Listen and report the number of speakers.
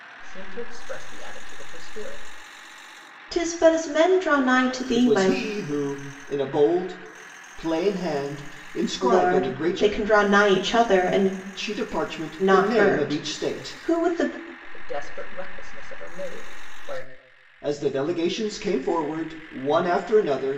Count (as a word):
three